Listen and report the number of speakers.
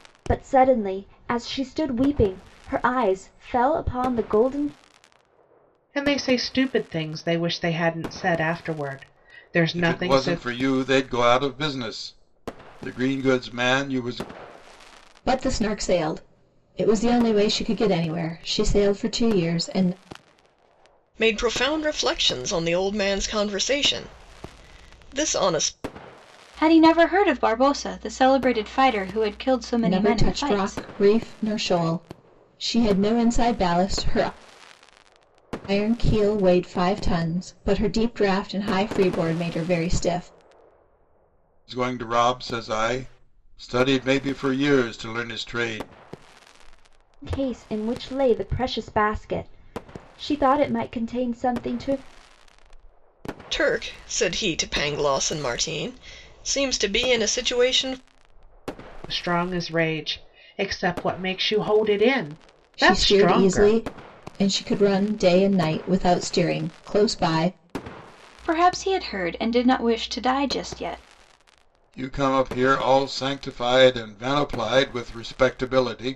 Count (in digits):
6